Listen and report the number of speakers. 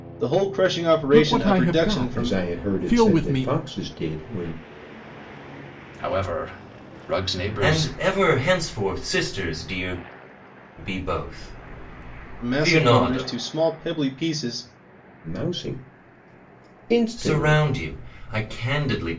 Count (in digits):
5